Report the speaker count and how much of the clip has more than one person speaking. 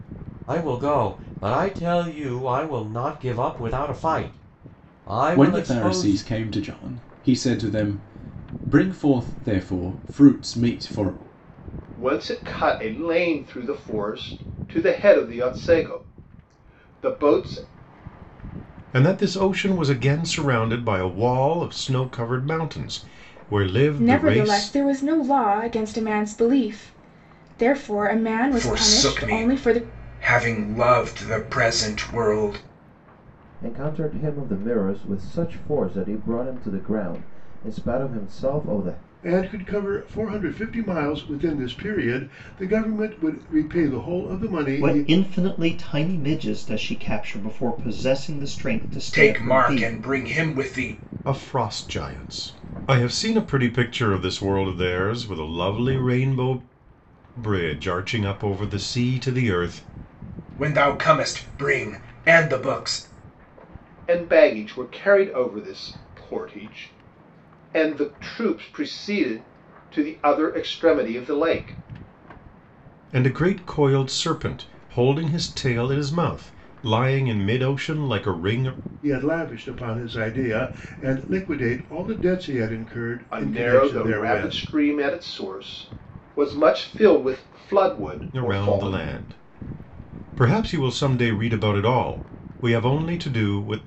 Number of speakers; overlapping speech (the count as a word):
nine, about 7%